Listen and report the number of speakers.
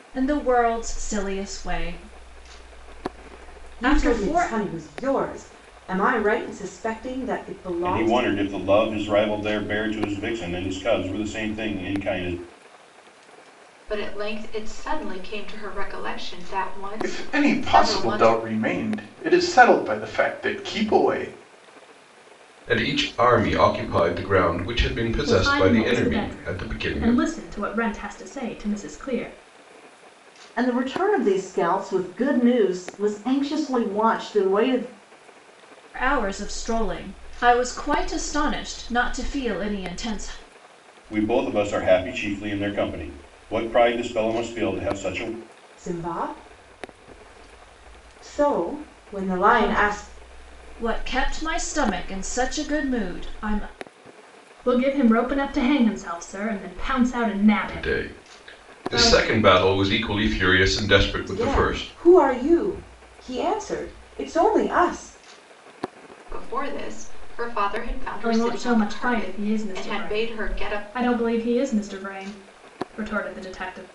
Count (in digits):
8